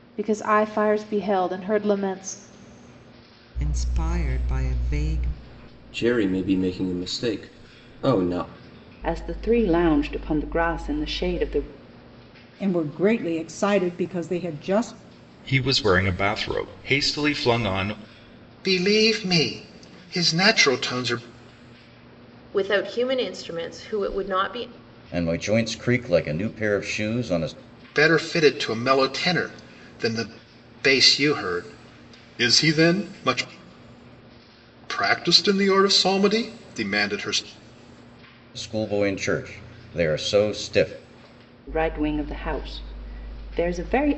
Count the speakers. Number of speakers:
9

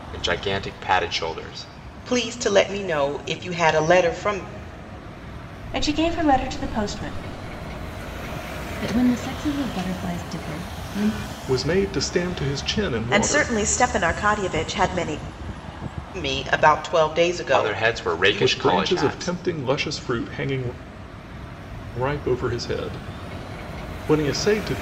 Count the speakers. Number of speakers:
6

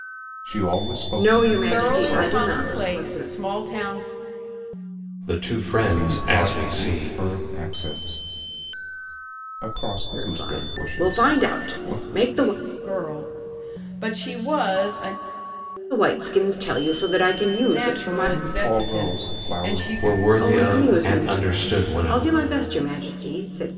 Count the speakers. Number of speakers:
4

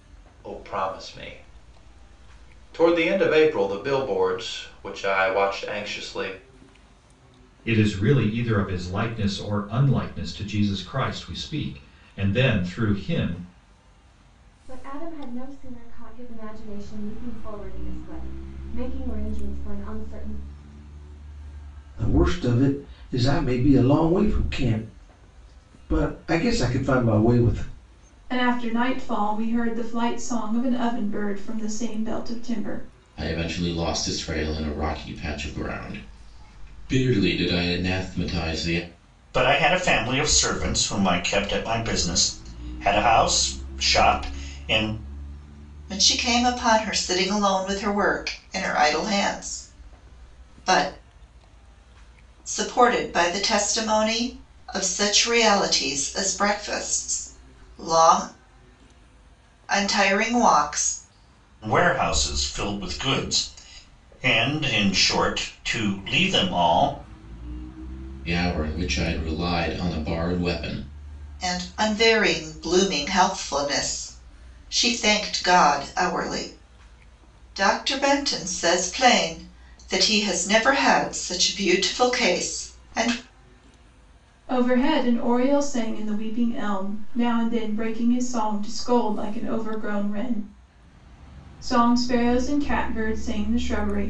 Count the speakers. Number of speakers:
8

